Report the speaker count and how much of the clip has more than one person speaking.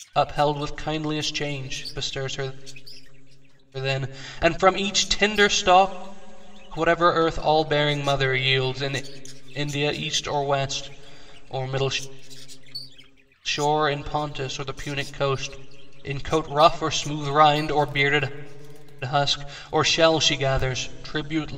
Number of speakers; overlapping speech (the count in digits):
1, no overlap